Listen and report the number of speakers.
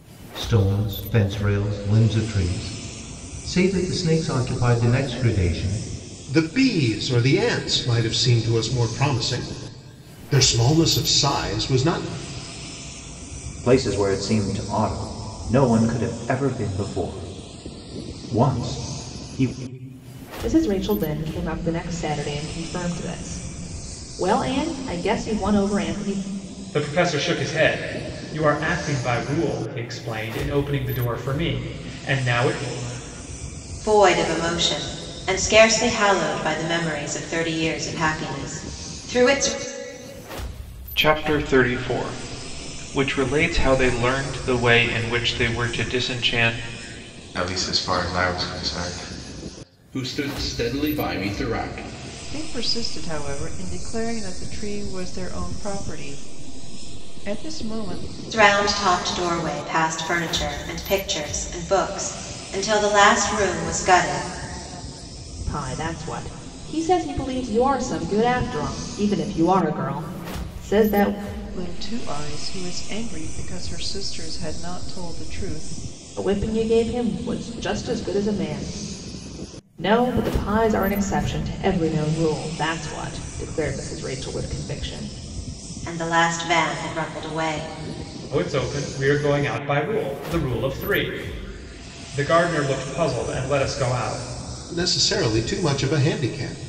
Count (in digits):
10